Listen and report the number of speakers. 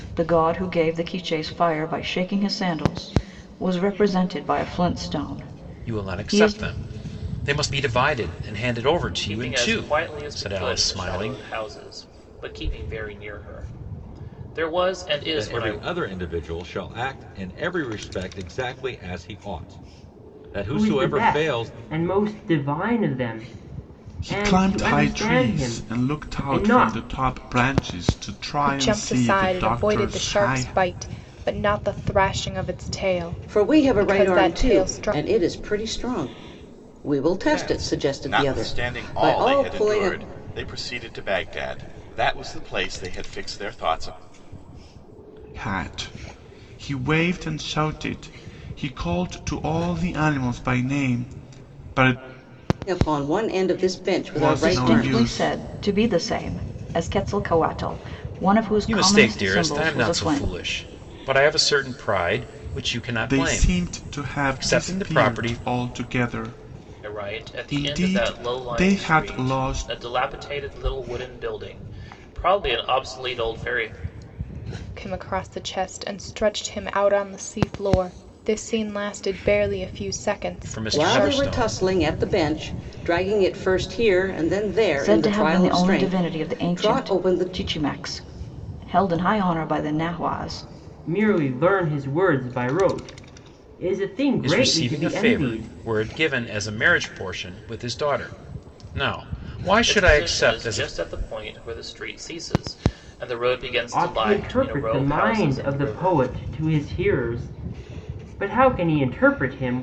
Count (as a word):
nine